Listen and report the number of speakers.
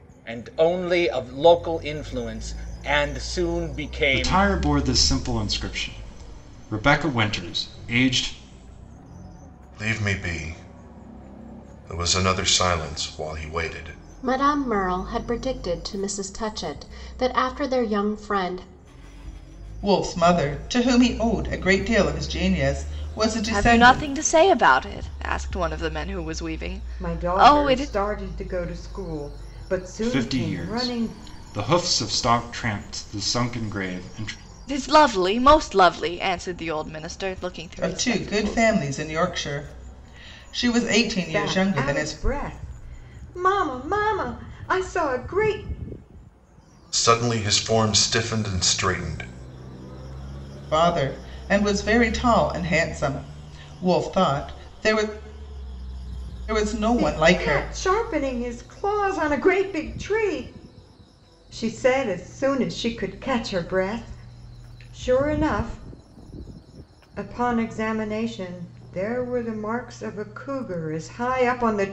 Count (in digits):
7